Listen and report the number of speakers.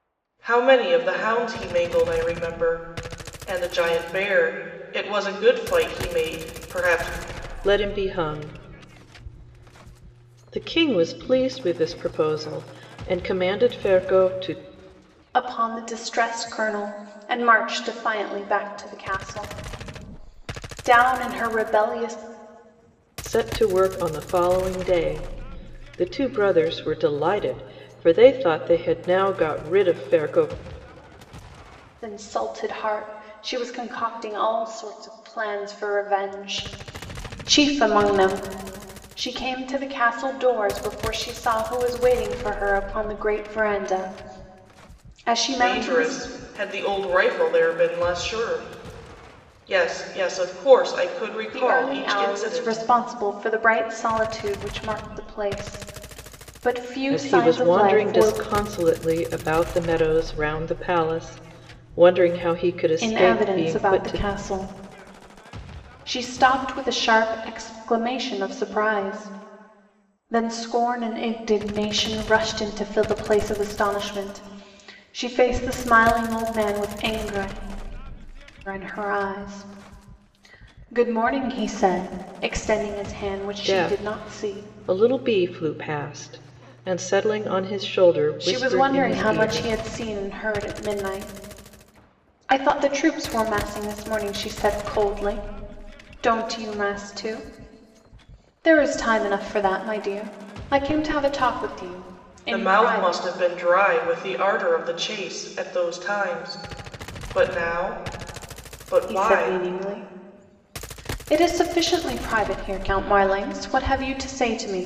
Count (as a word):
three